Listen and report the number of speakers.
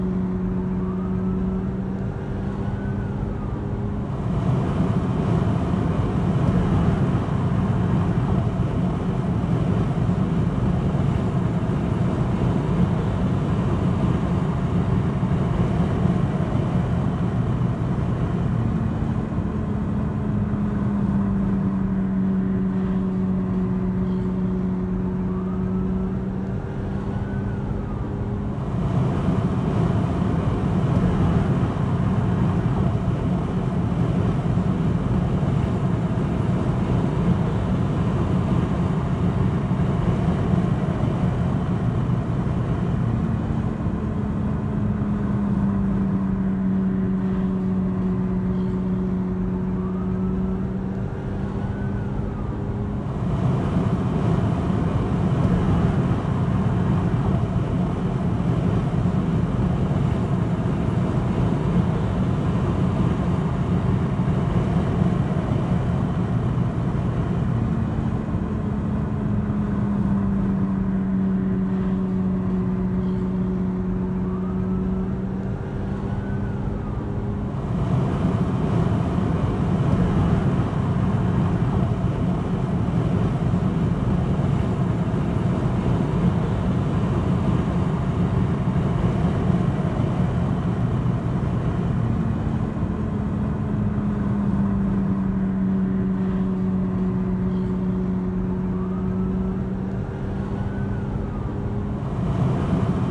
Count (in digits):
0